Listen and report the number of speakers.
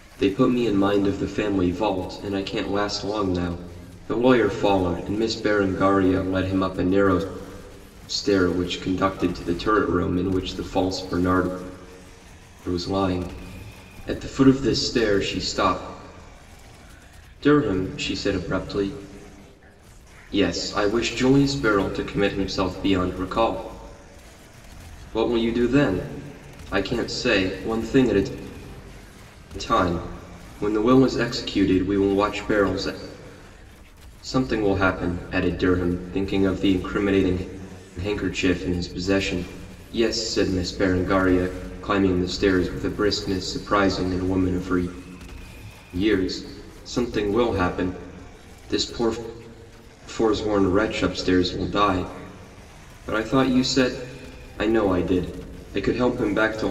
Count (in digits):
1